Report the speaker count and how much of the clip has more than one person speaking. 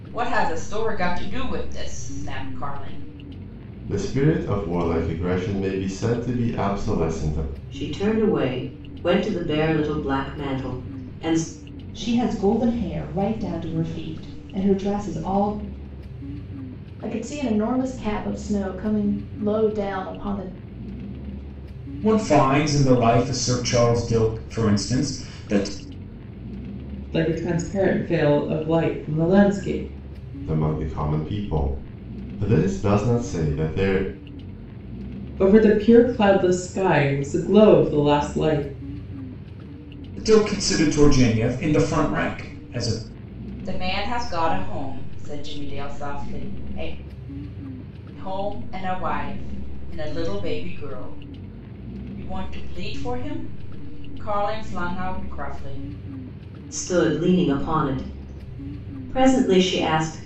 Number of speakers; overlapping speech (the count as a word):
seven, no overlap